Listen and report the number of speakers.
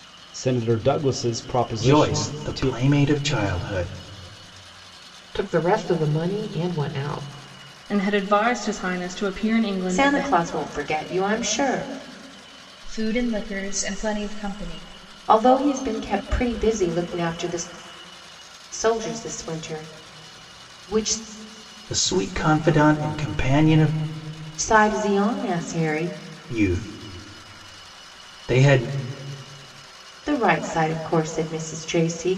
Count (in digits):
6